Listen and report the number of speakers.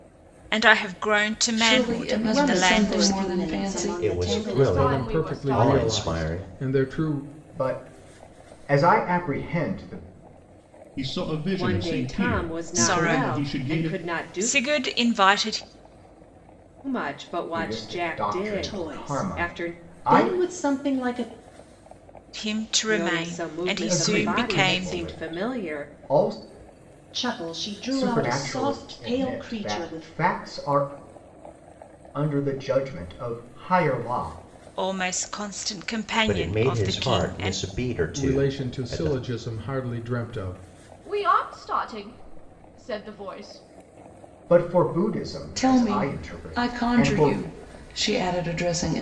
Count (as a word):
nine